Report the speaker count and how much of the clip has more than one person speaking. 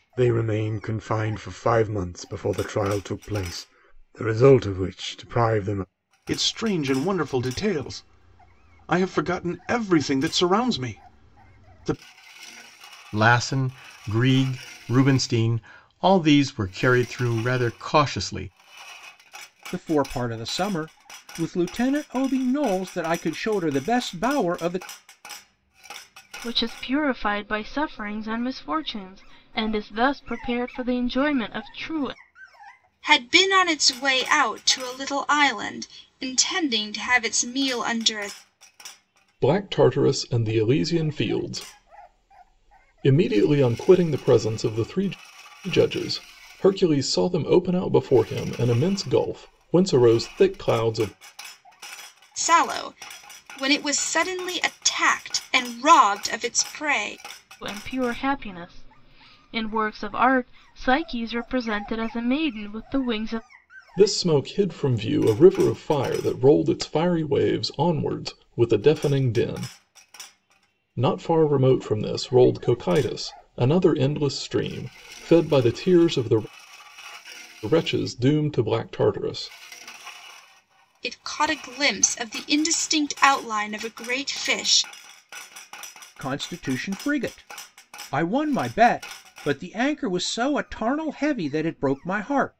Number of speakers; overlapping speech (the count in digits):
7, no overlap